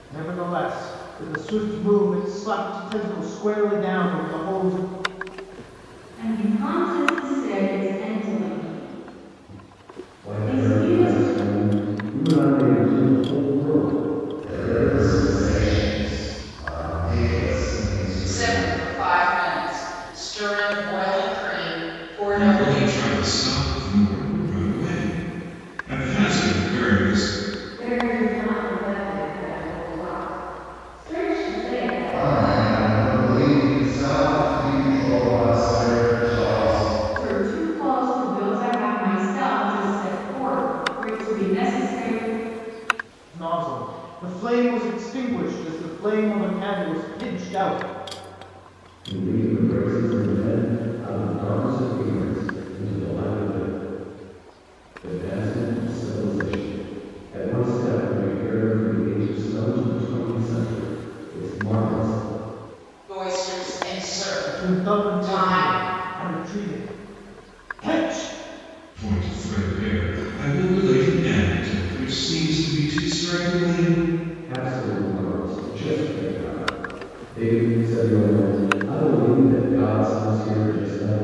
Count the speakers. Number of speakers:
seven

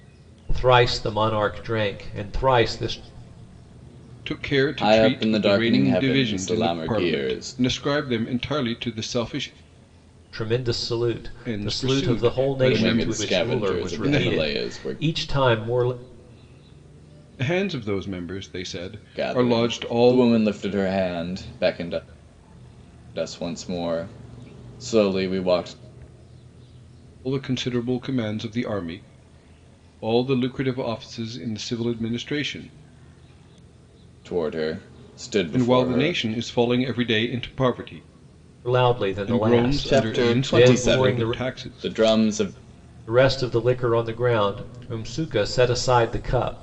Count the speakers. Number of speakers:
three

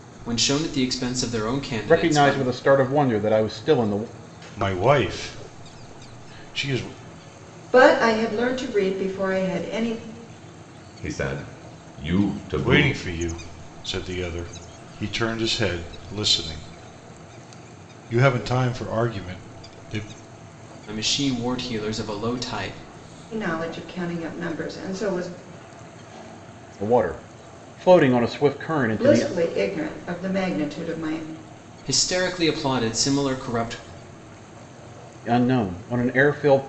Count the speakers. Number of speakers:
five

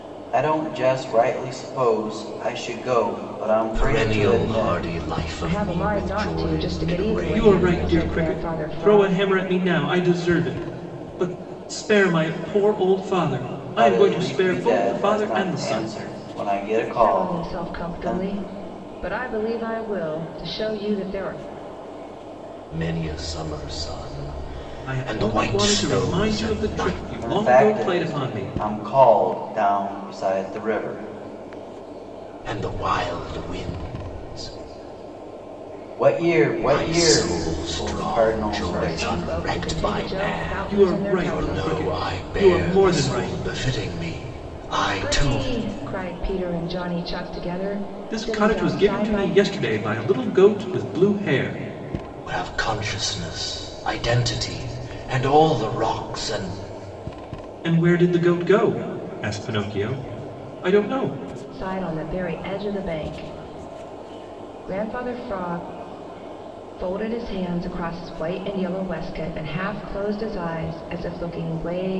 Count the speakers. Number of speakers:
four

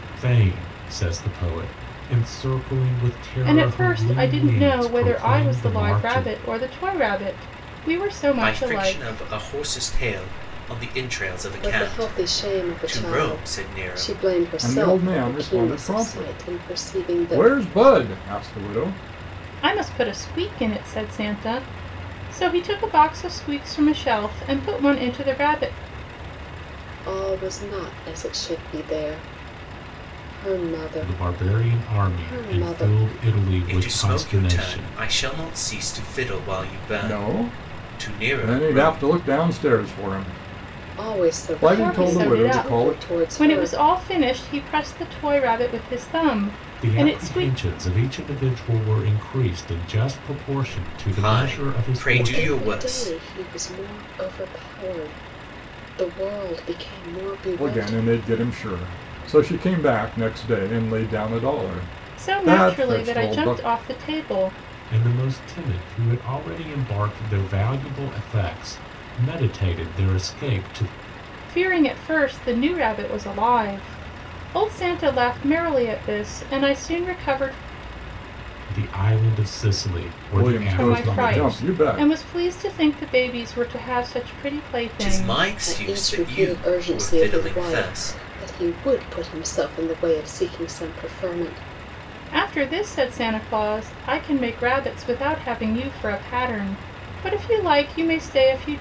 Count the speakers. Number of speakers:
five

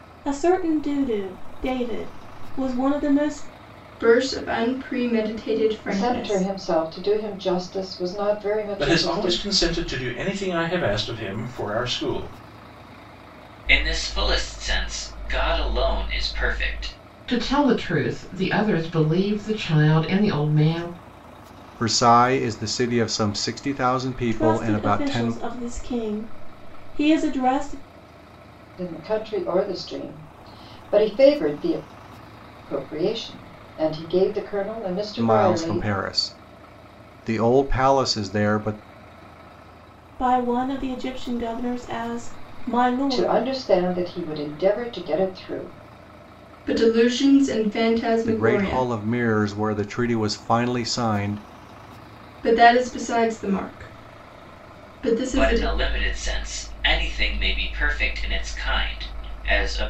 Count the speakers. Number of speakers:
seven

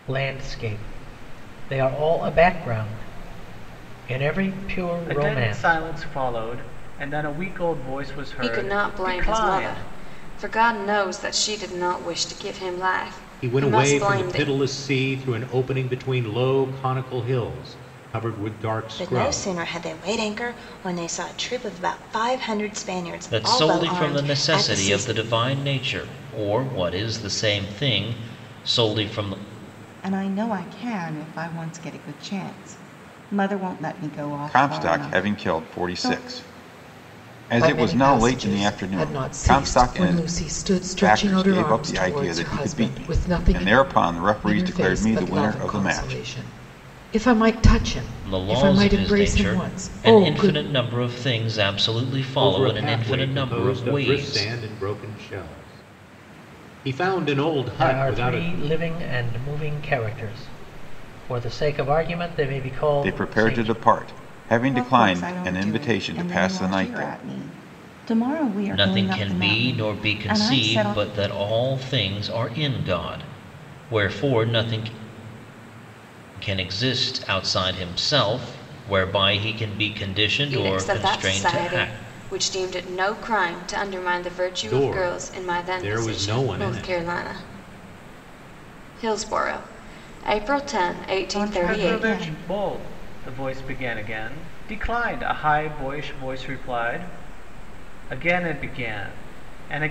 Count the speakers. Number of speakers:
nine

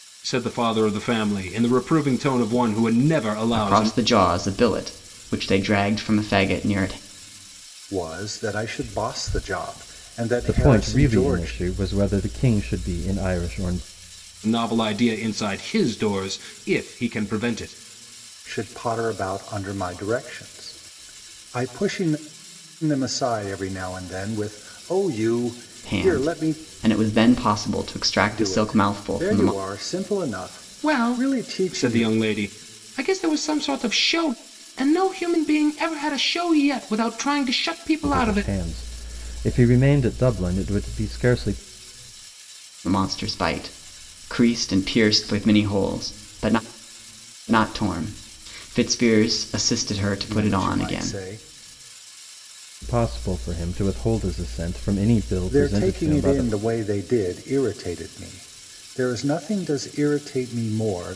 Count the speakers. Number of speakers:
four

